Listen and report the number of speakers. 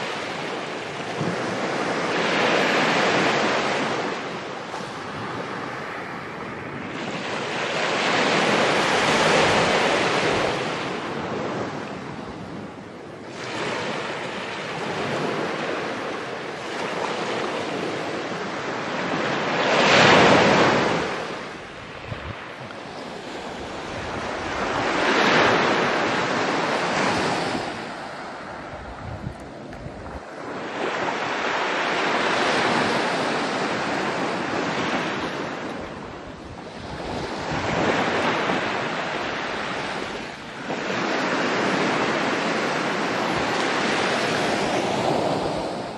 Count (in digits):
0